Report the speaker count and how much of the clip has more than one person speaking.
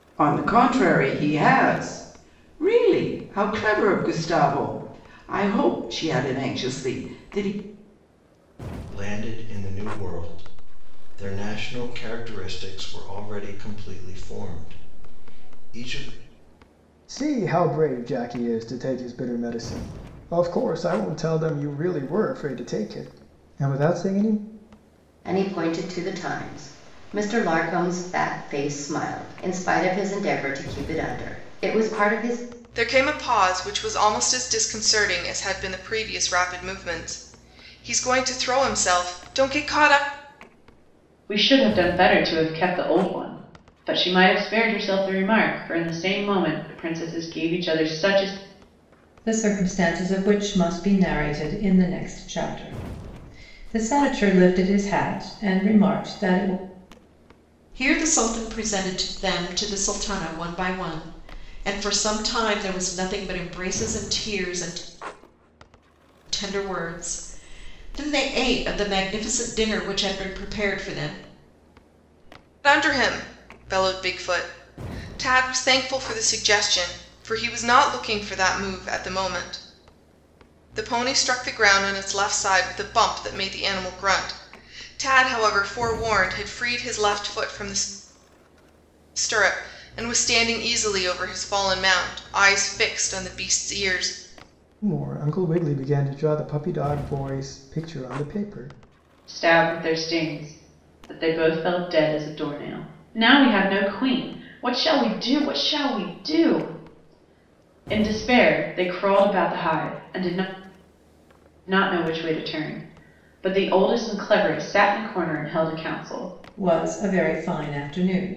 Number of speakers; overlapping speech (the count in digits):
8, no overlap